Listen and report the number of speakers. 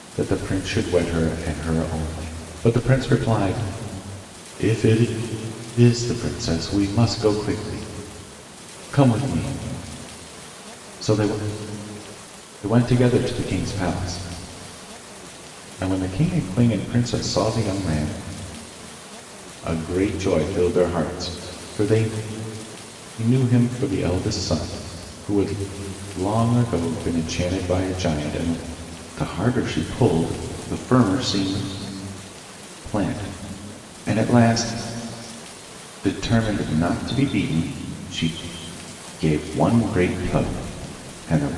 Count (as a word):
one